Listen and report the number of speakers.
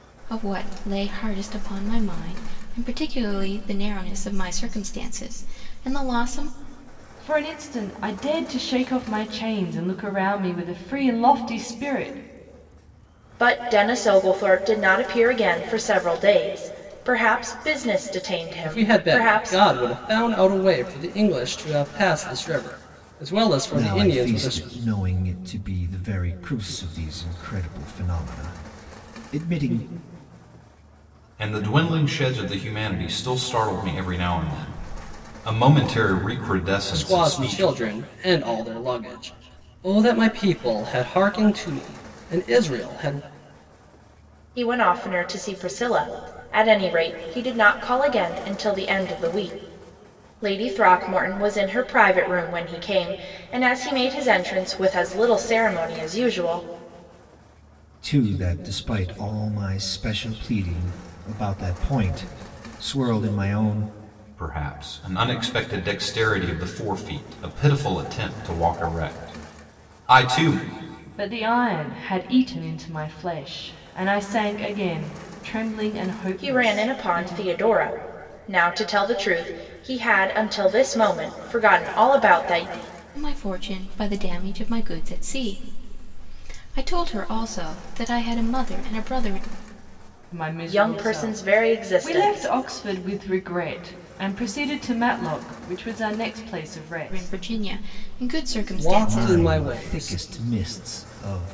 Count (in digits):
6